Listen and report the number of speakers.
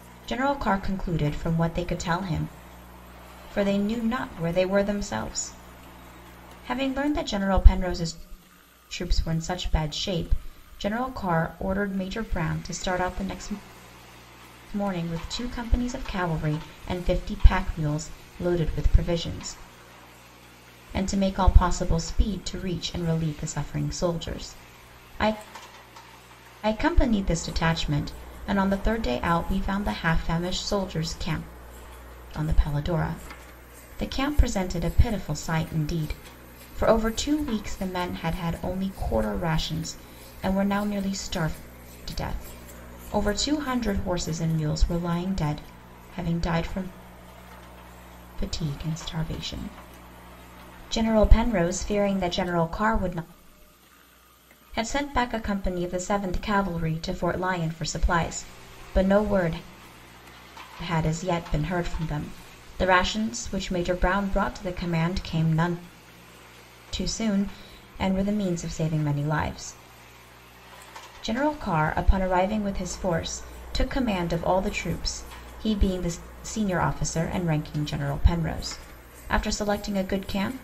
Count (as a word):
one